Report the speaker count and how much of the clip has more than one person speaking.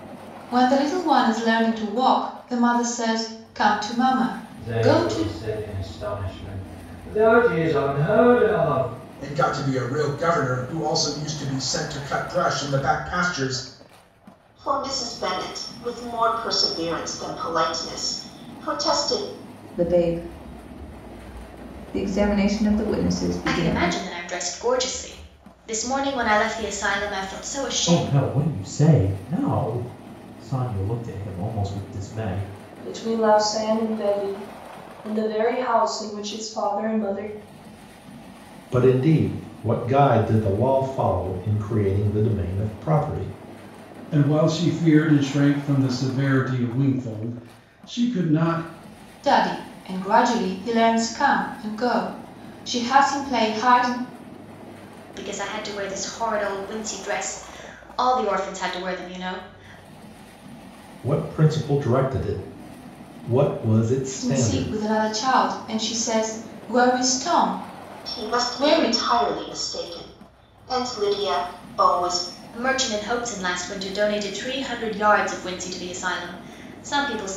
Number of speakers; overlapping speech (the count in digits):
10, about 4%